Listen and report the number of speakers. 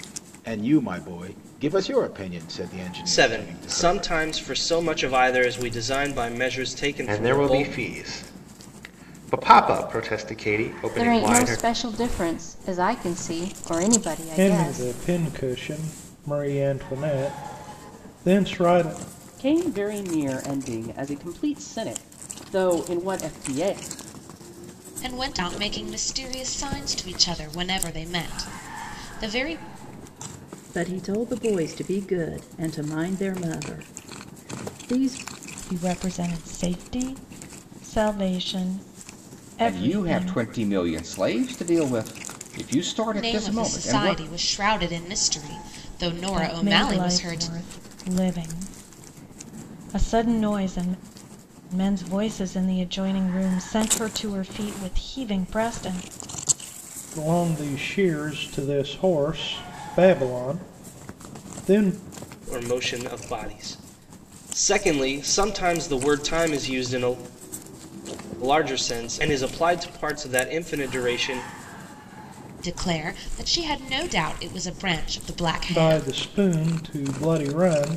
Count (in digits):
10